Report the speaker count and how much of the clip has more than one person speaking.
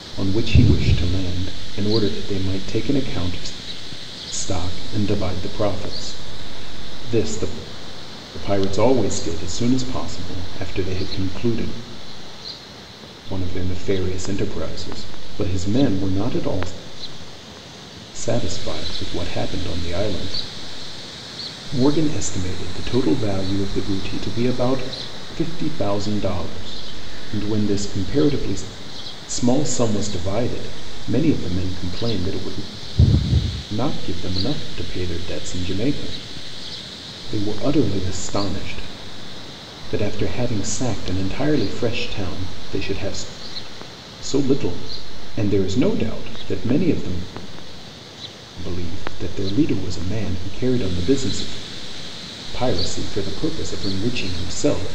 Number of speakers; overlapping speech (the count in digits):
1, no overlap